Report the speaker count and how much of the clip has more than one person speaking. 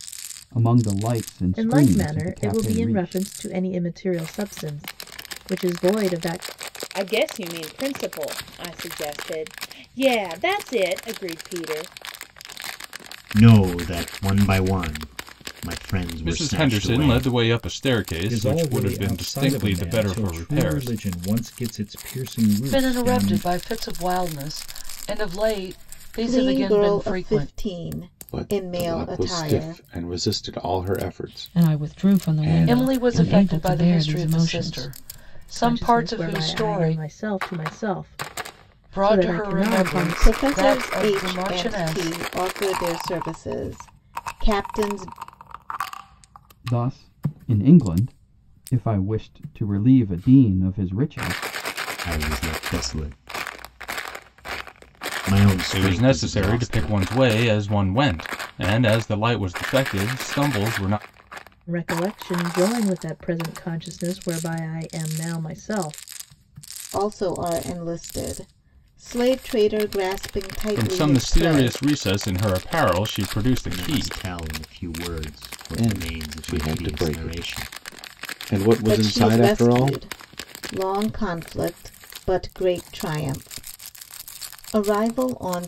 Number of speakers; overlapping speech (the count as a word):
ten, about 28%